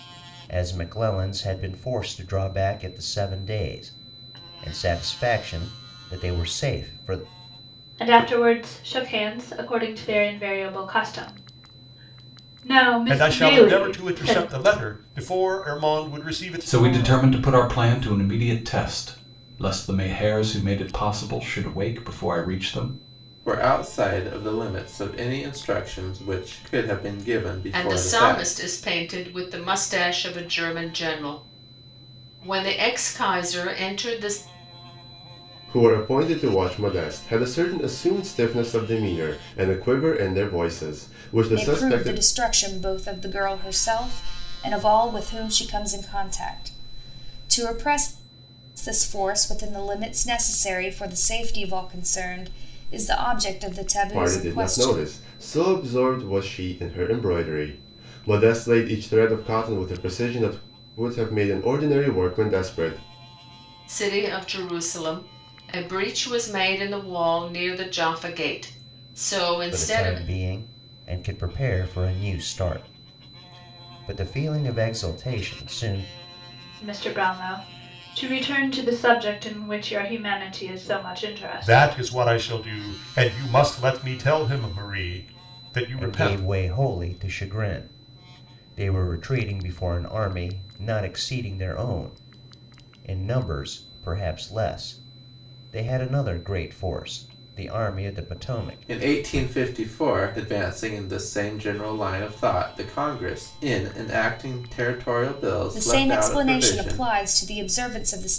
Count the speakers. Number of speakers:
eight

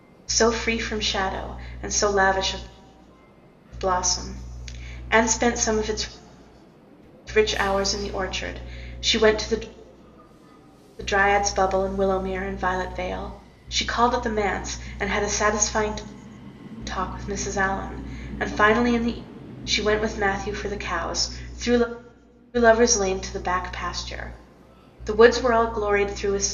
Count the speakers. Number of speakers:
one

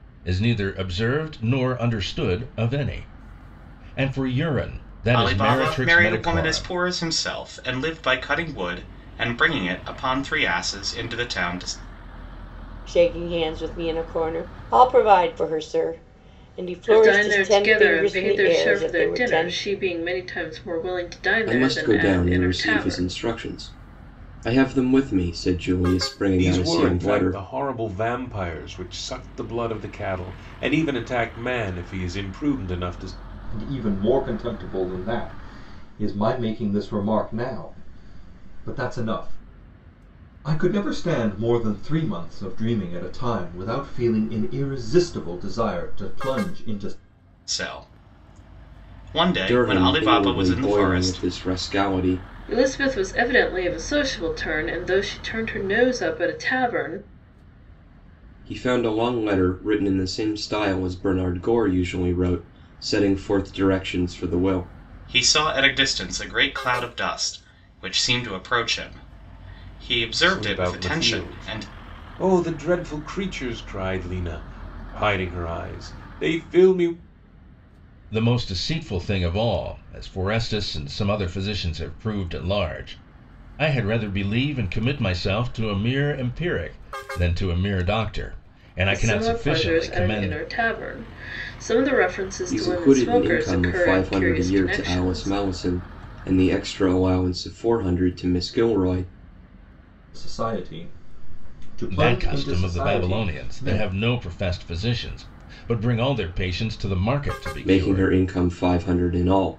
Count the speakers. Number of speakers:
seven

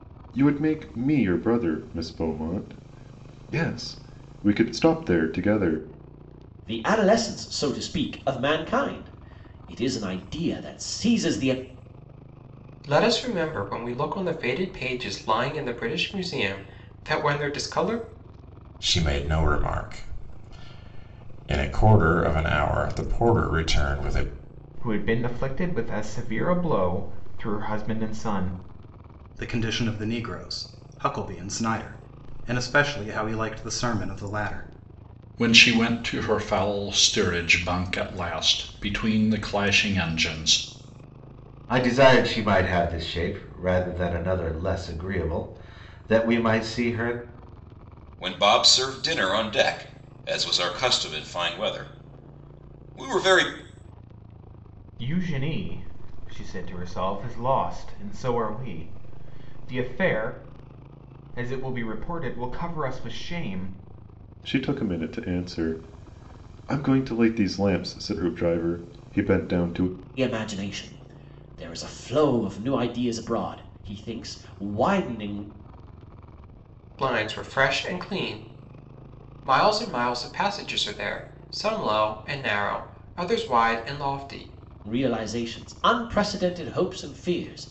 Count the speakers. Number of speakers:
nine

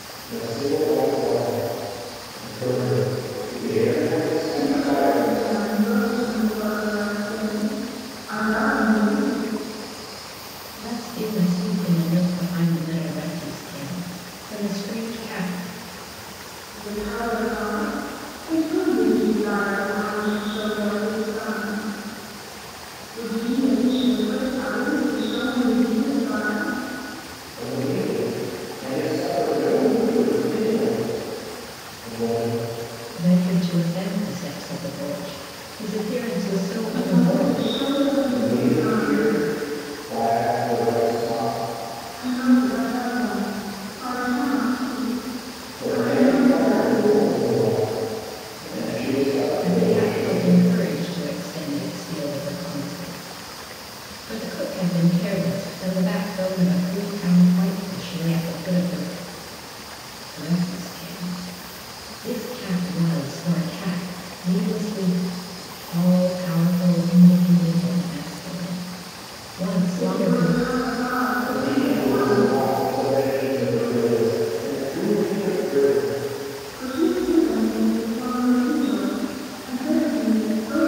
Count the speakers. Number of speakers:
three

